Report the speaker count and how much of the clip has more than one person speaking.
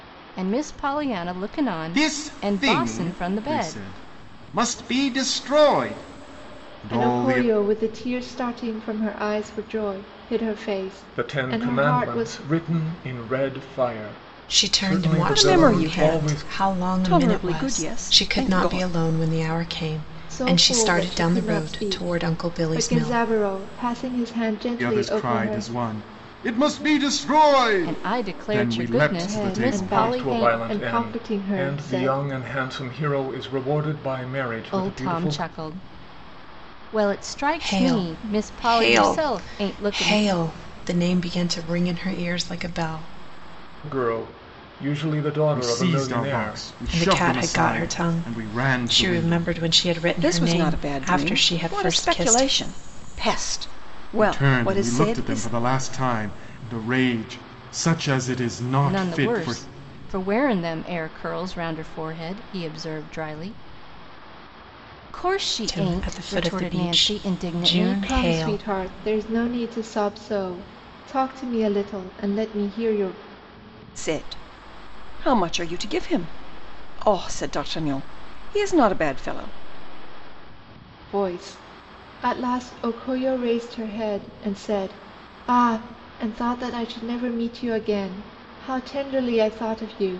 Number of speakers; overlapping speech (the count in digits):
6, about 34%